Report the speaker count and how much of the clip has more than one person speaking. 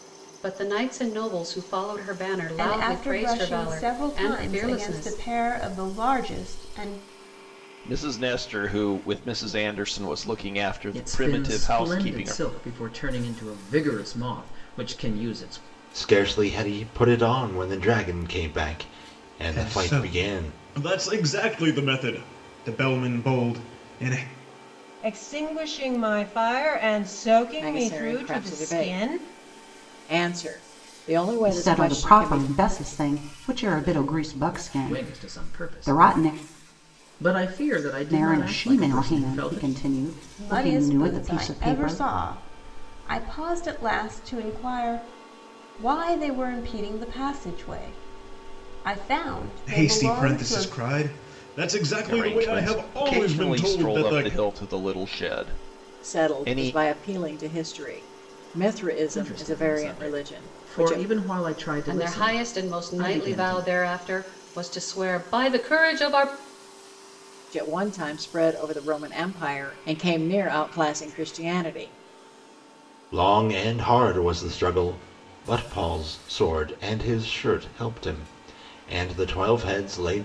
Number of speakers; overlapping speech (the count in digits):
9, about 25%